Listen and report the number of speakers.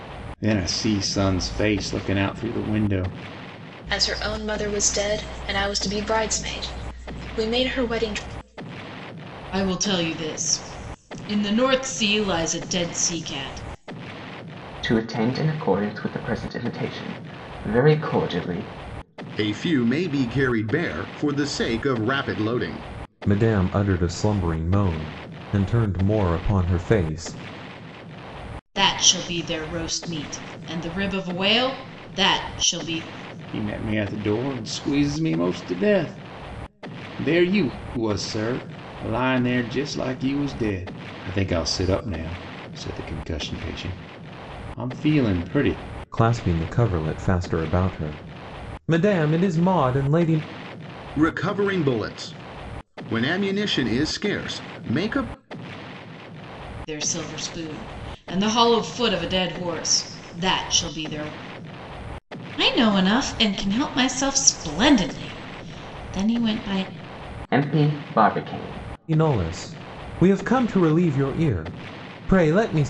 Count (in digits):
6